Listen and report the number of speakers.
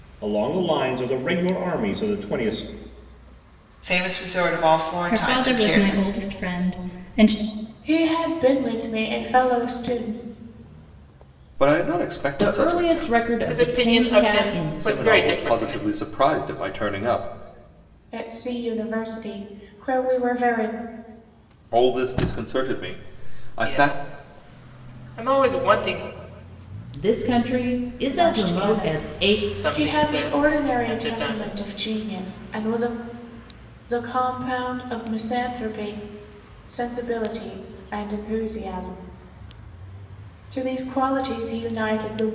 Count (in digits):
7